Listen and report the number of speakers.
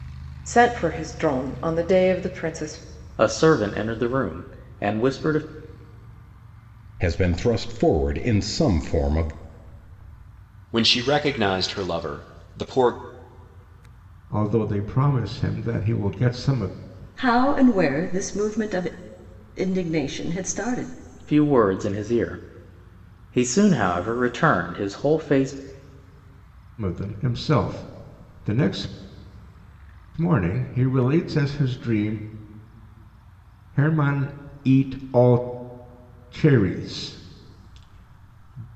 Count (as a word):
six